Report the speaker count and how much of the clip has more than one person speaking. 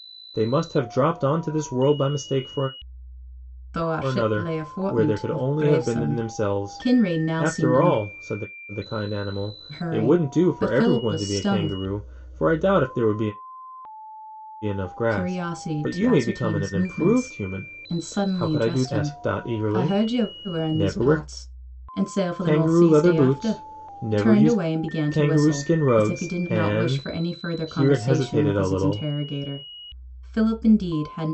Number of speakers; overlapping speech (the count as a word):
two, about 56%